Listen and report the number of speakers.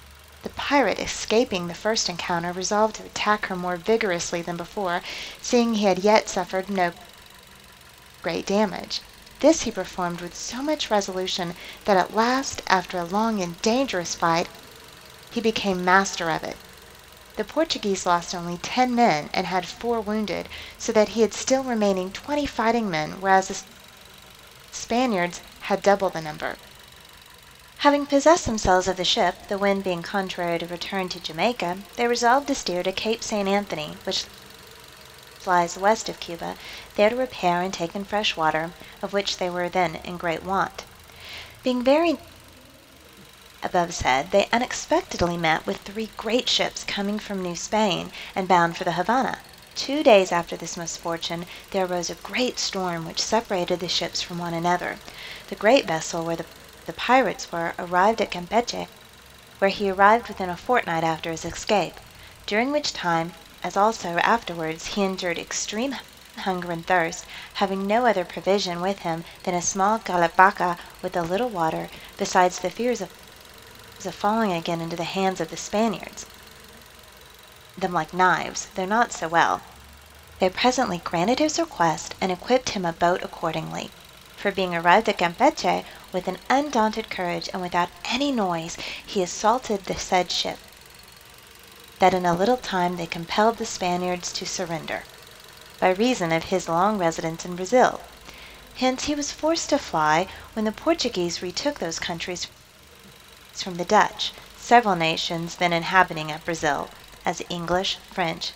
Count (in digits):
1